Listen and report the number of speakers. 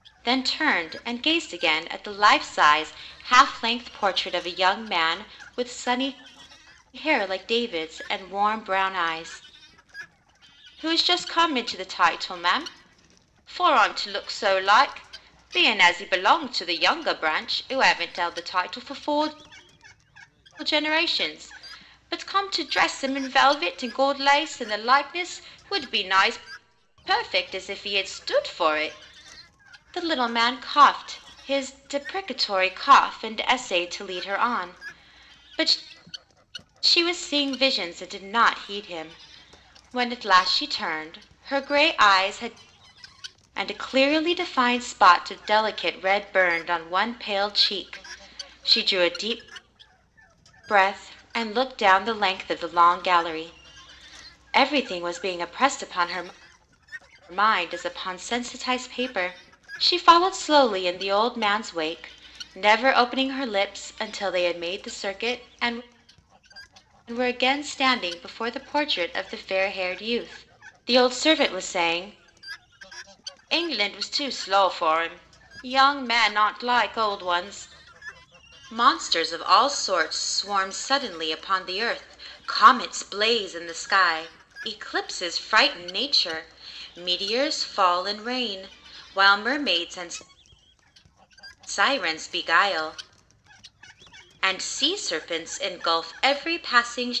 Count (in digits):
1